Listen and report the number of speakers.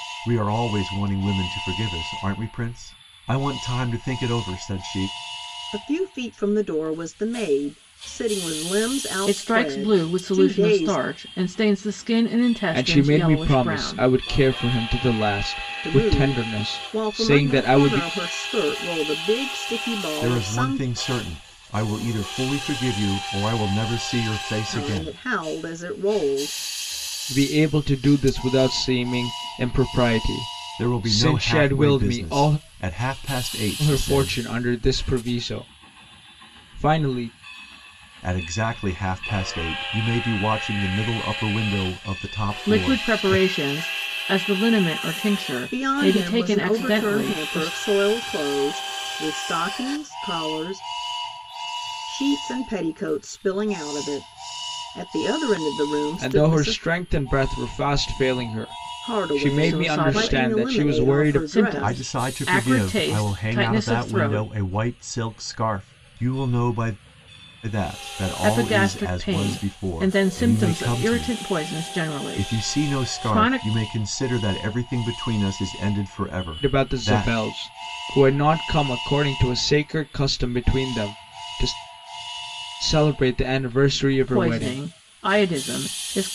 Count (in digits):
4